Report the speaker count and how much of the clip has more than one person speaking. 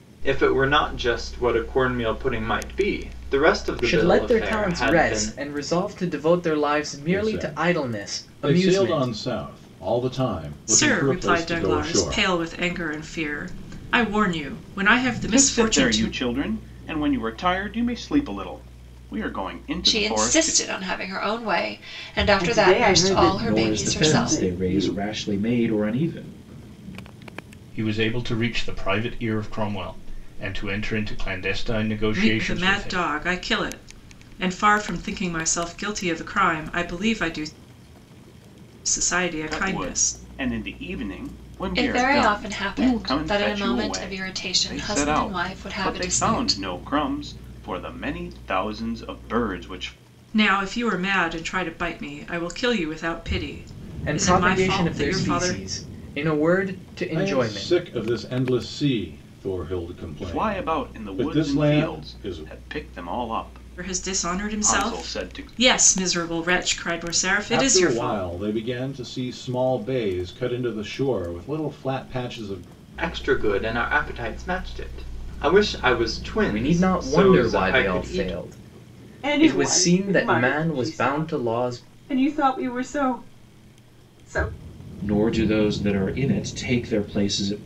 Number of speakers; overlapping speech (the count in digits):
9, about 31%